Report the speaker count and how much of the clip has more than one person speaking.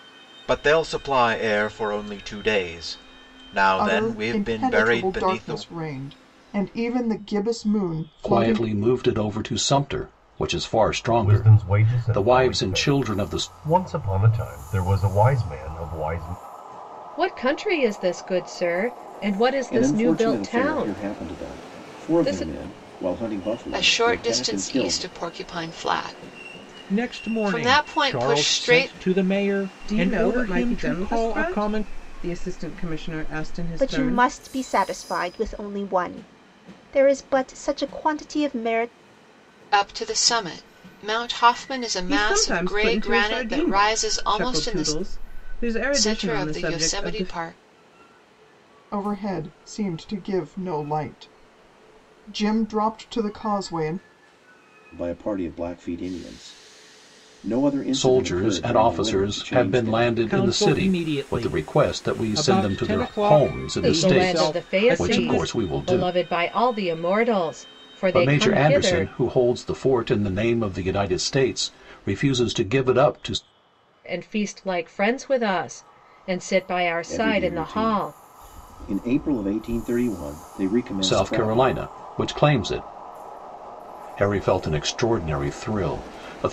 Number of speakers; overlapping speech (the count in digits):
10, about 33%